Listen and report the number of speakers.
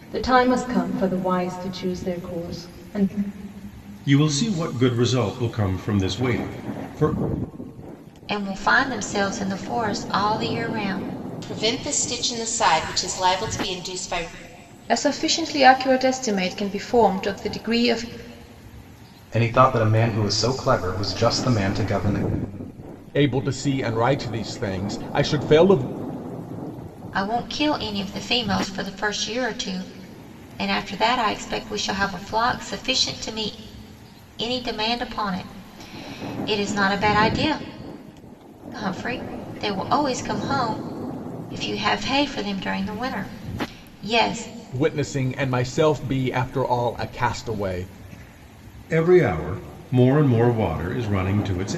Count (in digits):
7